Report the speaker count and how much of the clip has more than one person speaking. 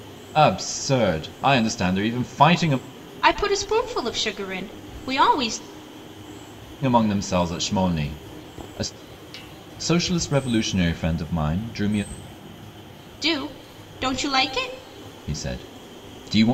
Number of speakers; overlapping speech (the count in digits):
2, no overlap